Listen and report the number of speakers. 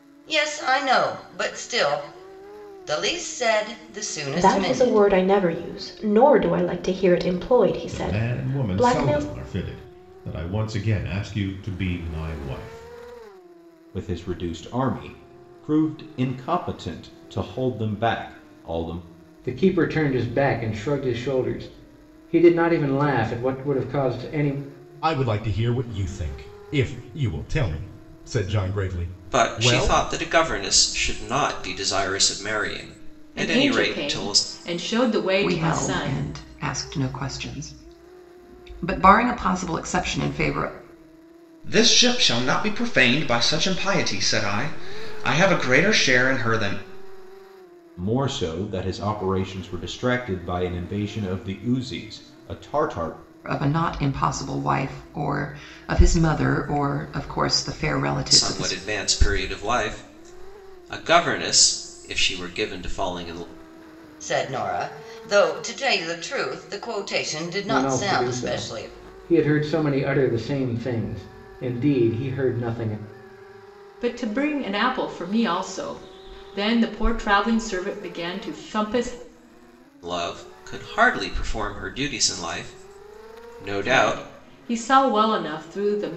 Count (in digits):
10